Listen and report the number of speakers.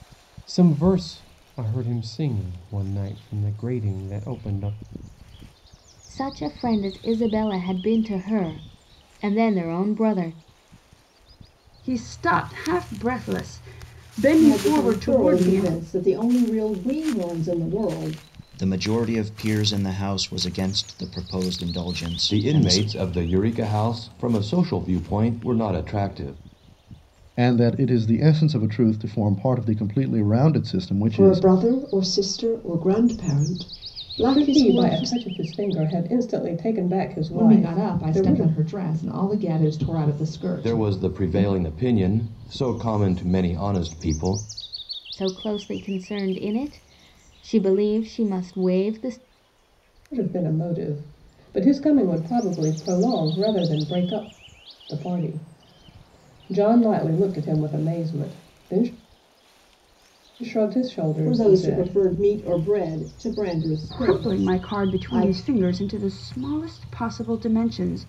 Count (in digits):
10